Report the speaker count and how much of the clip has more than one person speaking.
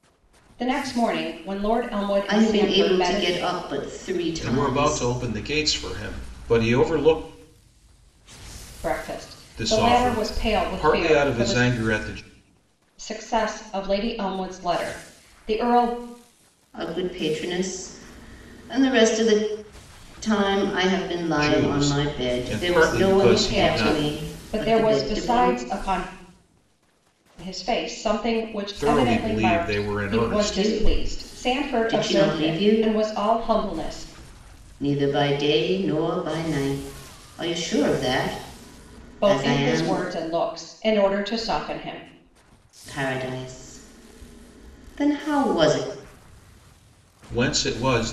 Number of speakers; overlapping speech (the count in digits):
3, about 27%